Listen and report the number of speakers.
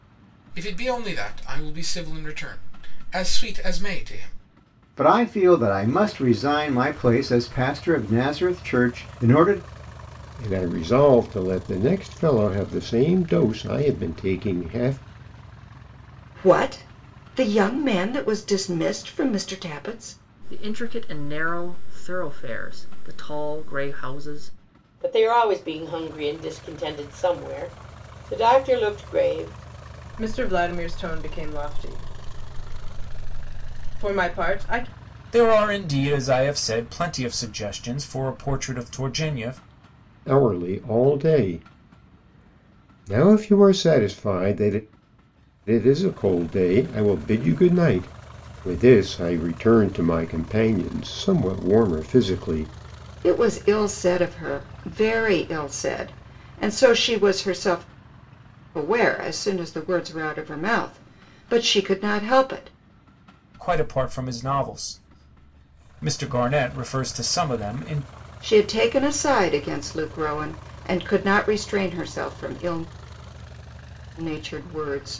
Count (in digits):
8